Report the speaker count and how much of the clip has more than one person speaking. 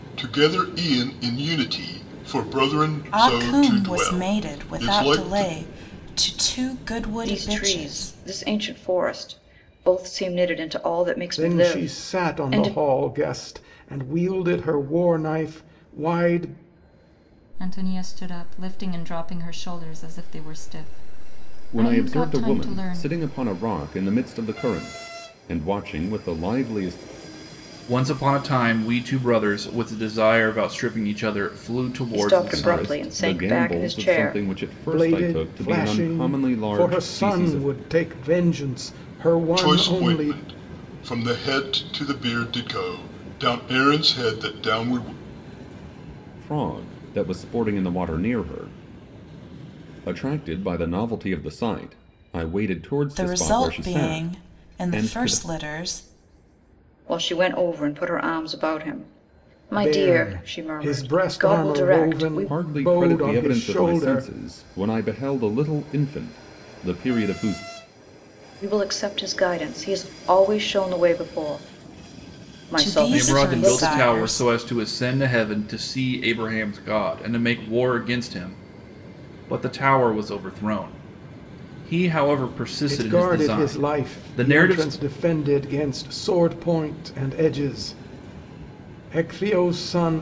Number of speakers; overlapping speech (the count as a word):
seven, about 26%